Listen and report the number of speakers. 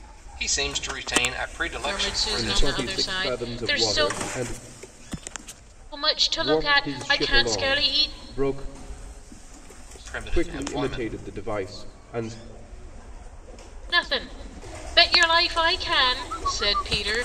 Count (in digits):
3